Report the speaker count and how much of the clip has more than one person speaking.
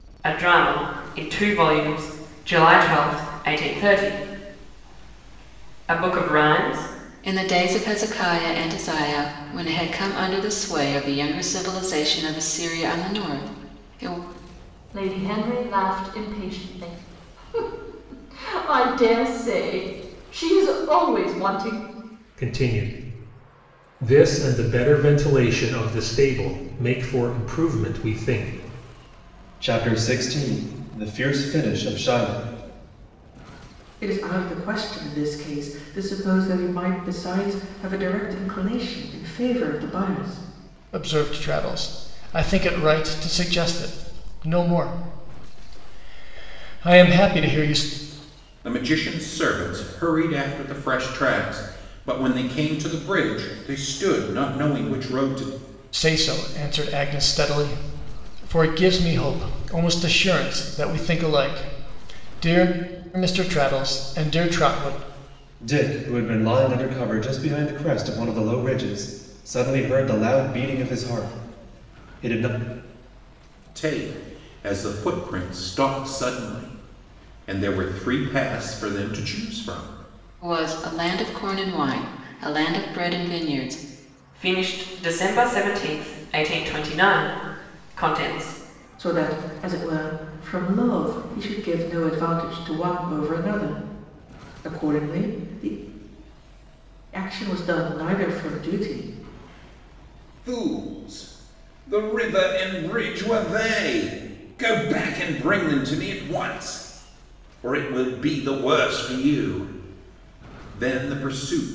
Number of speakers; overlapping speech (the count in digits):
8, no overlap